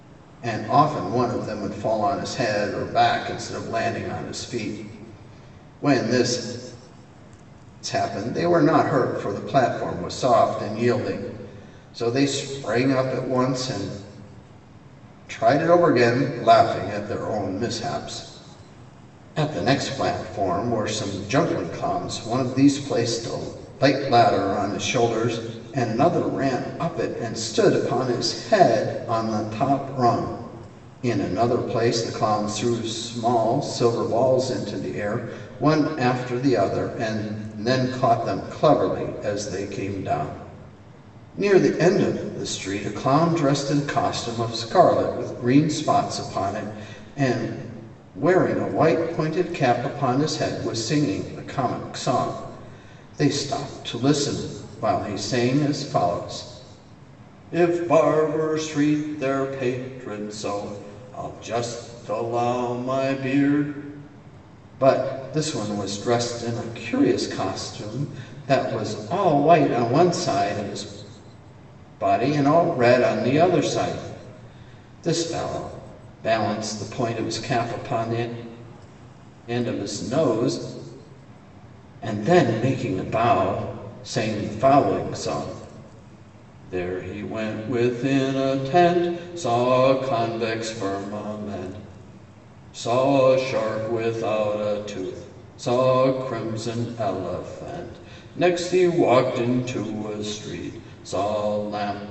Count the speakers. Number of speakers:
one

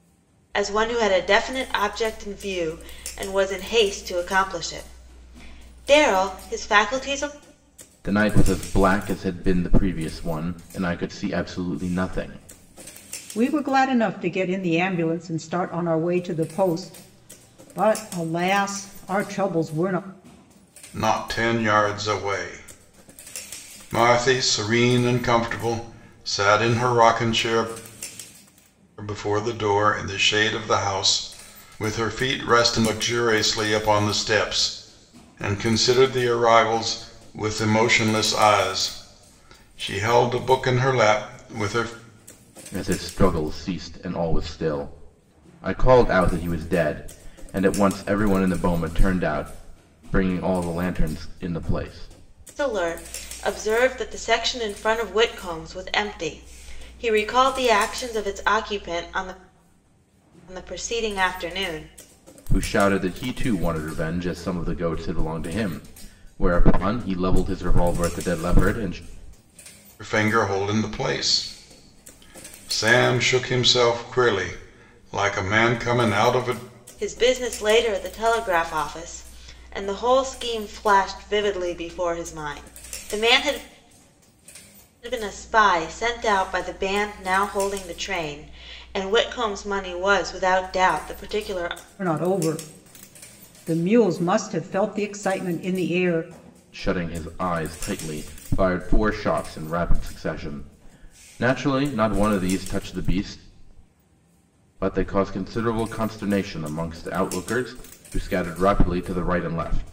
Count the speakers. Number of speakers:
four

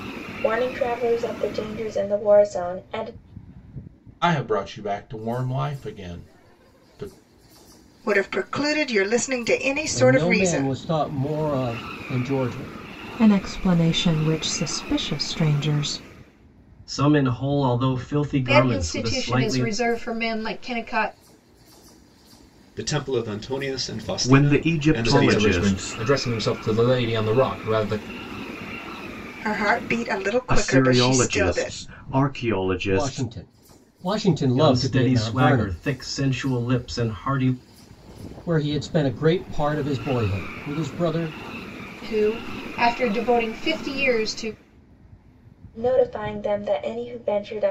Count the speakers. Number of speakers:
ten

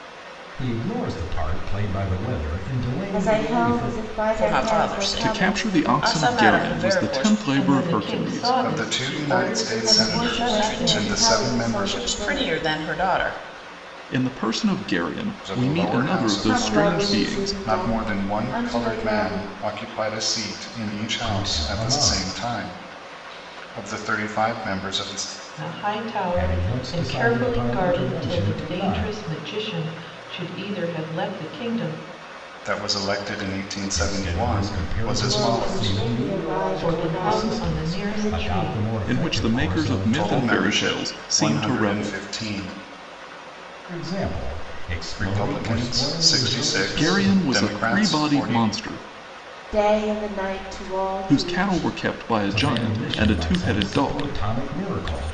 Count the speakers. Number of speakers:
six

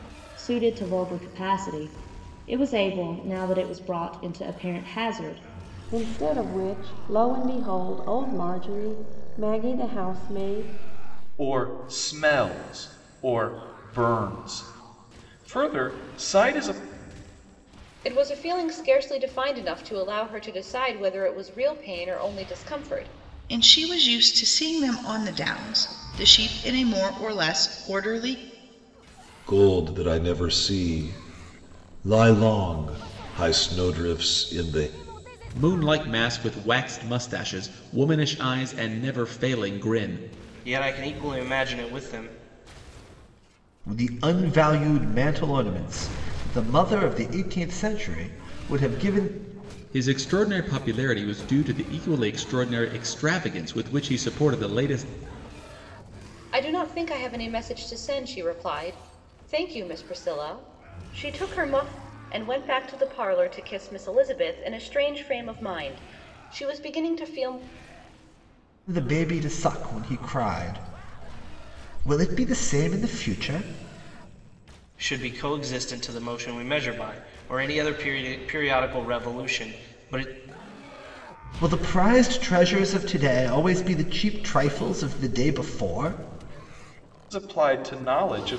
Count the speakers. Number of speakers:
nine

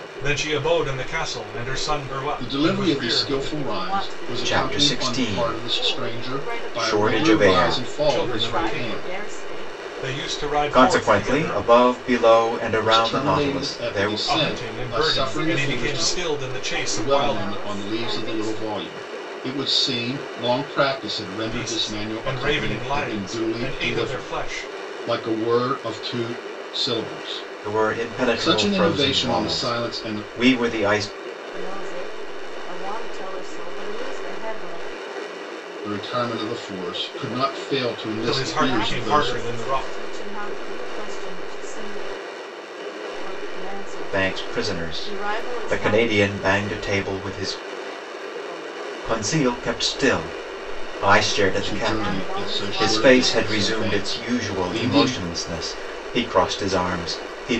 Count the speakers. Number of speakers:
four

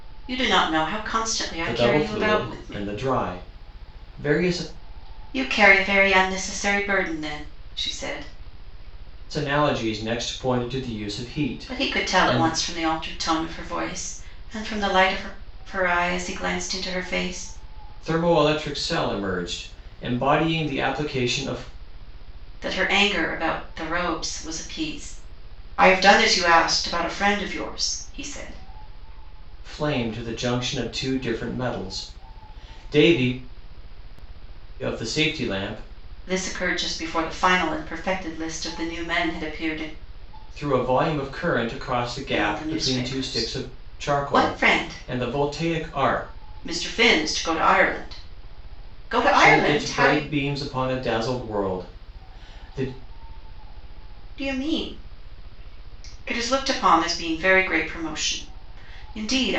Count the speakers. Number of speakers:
two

